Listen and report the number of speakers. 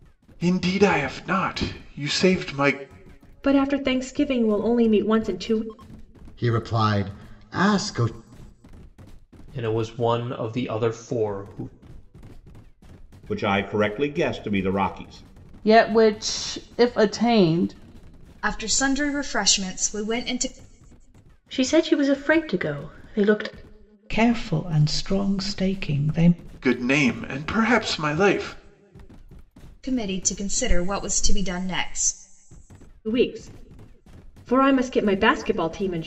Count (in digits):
9